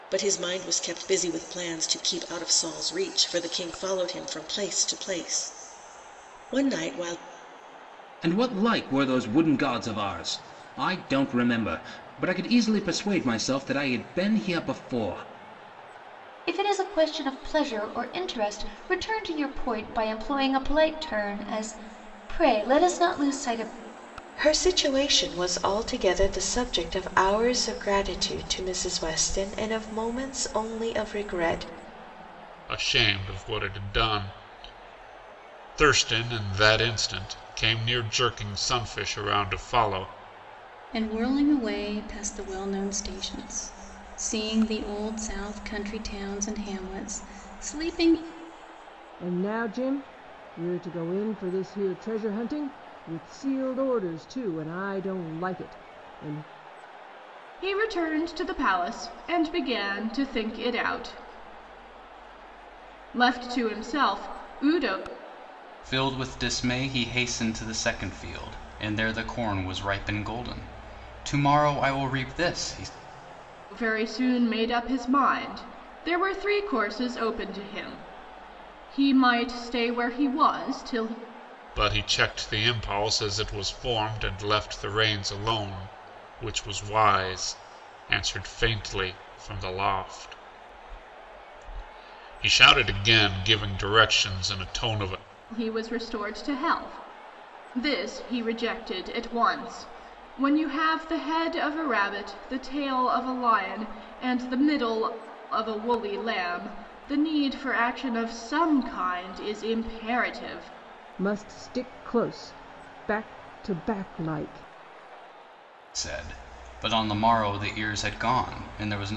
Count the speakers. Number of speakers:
9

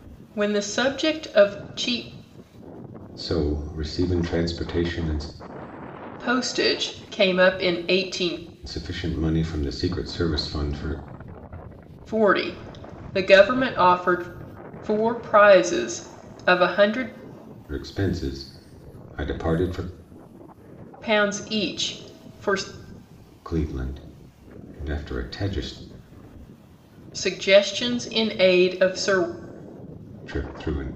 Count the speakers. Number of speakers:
2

